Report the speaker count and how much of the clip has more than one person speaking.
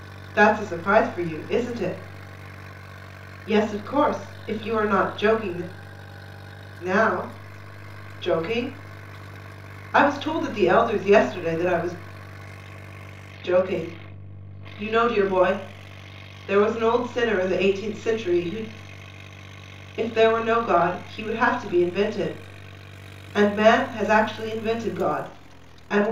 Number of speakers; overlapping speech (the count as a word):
one, no overlap